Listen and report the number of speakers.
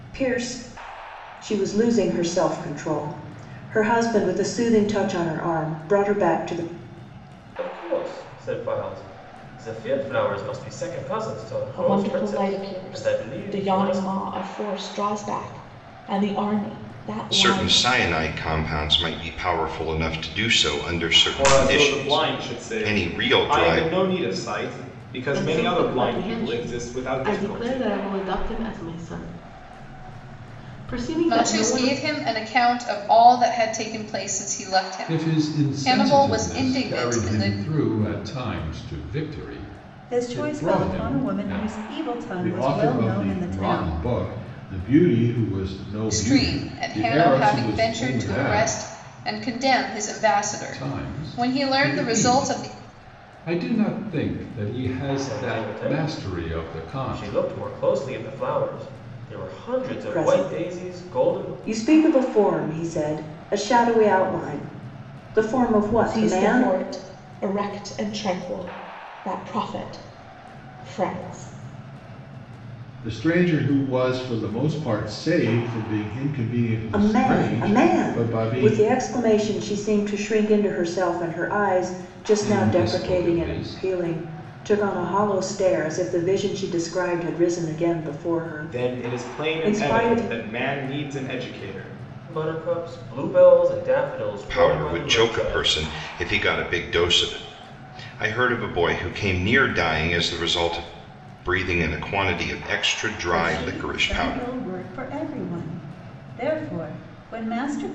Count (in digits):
10